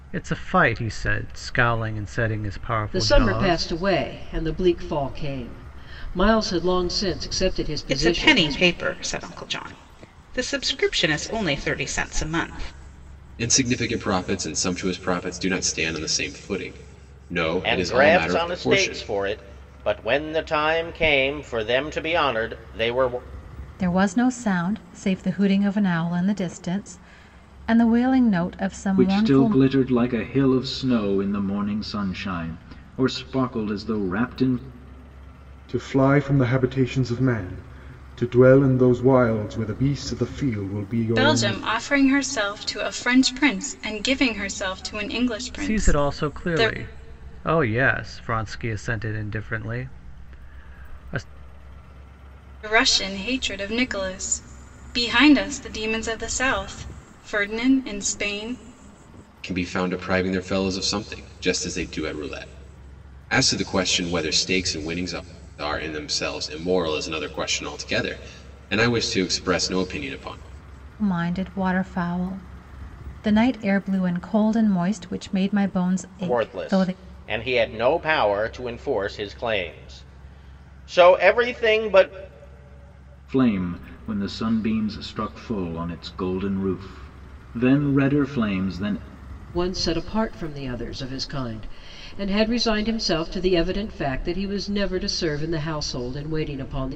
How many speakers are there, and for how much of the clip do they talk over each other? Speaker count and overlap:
9, about 6%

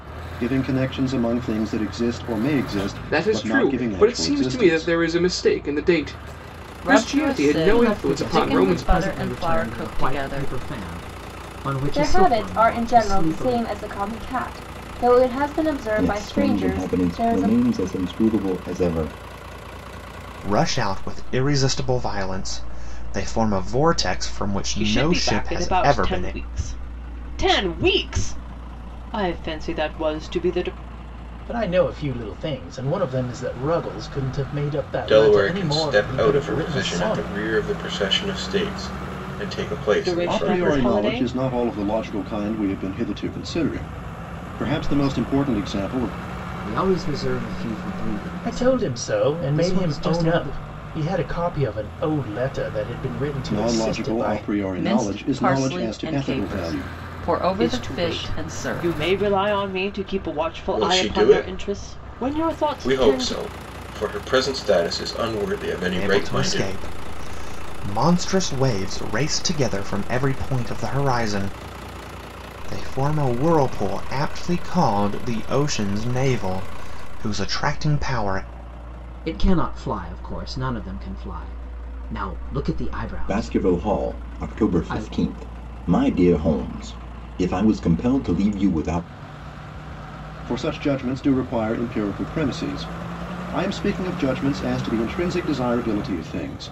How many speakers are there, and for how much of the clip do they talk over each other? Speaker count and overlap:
10, about 29%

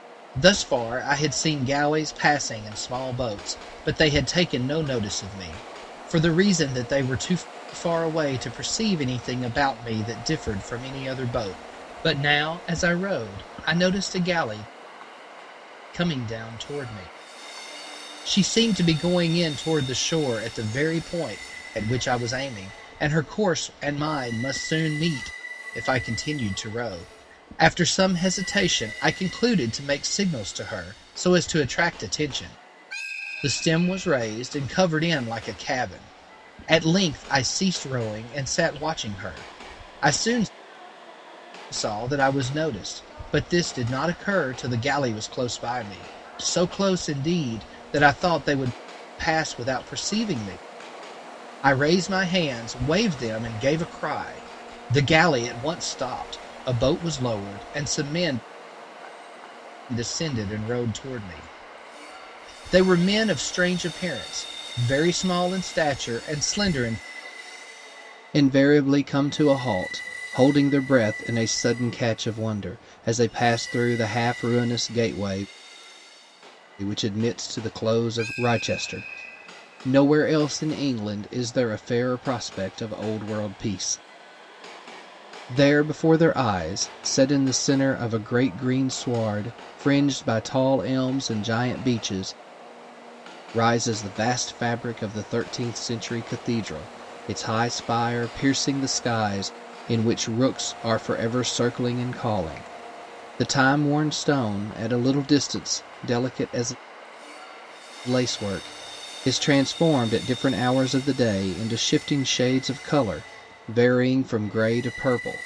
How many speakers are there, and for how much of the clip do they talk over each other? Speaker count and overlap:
1, no overlap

